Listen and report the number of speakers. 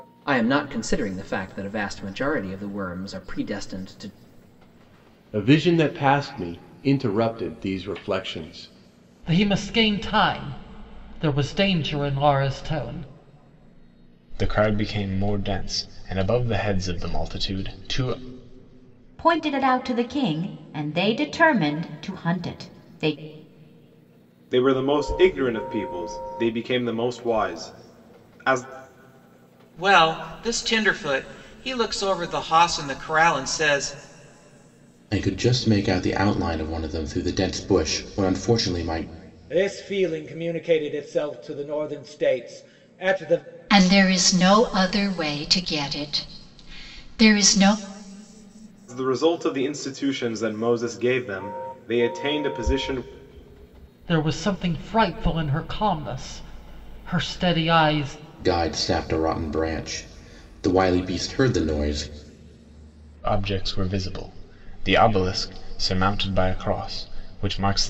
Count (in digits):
10